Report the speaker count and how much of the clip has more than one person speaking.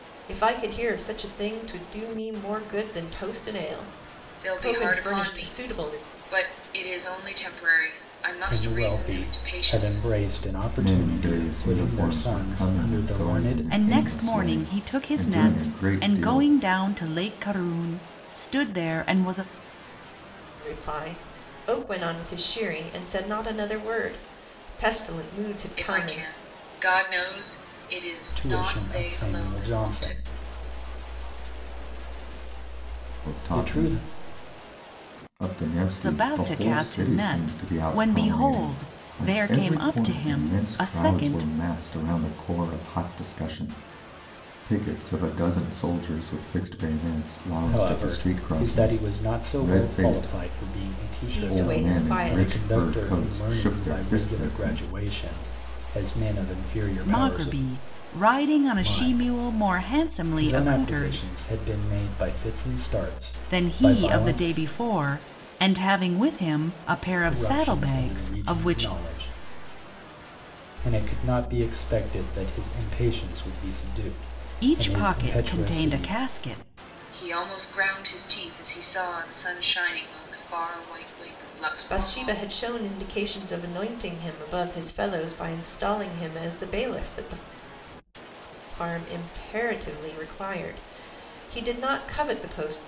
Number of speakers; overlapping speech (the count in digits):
5, about 34%